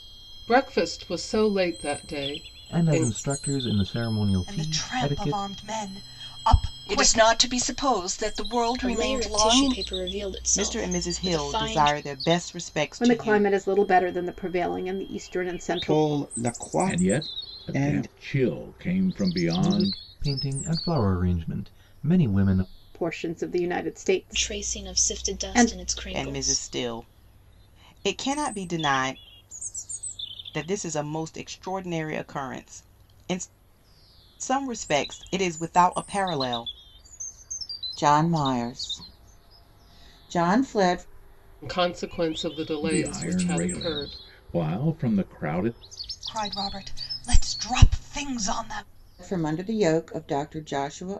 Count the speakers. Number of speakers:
nine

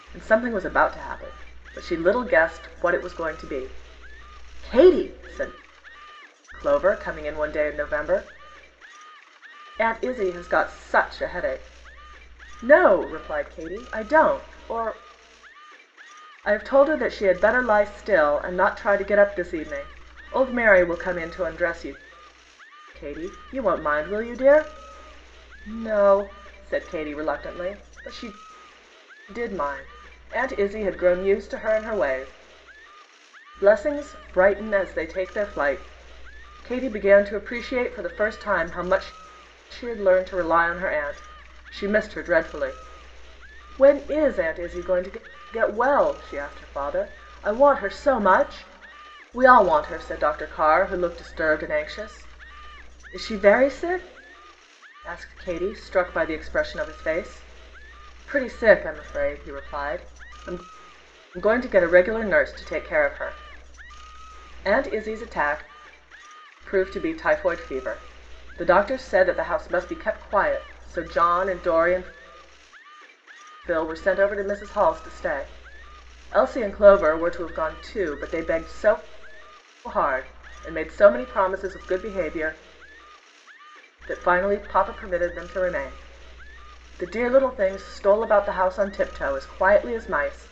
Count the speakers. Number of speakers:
one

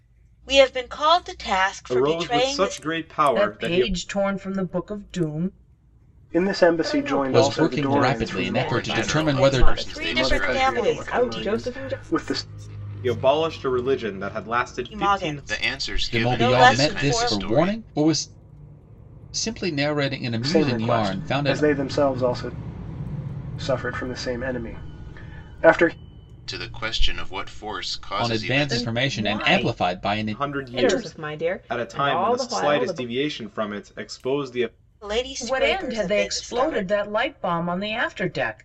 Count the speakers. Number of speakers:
seven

